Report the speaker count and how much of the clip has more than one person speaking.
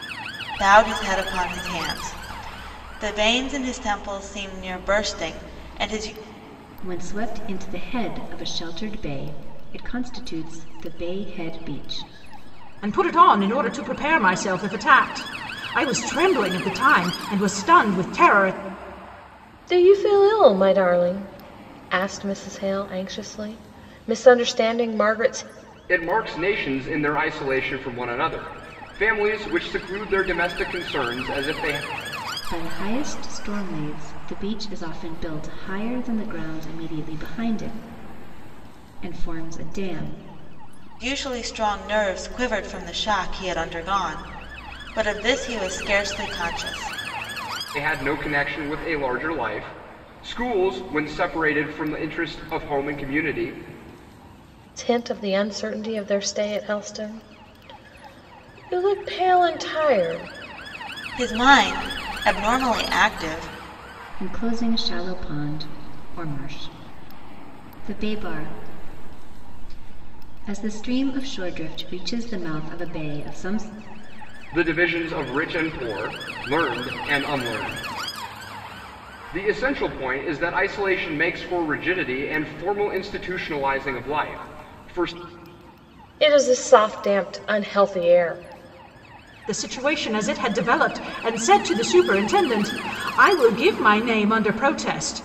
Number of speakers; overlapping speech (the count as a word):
five, no overlap